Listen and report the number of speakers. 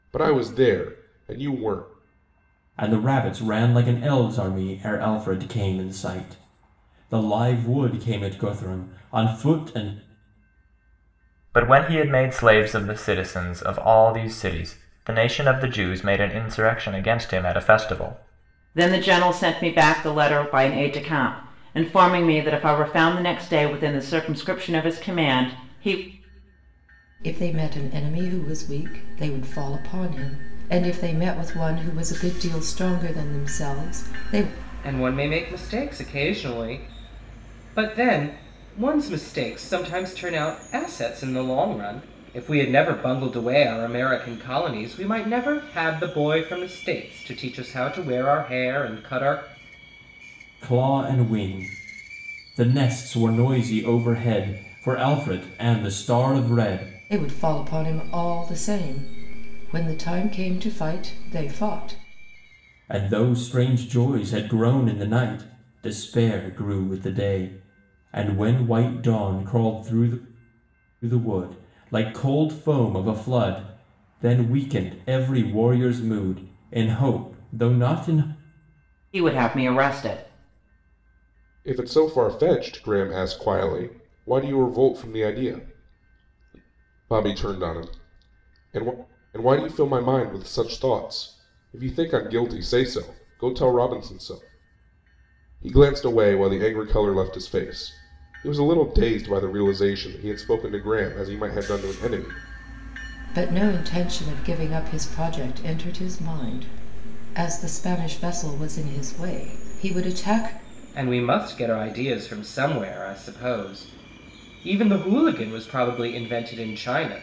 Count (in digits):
6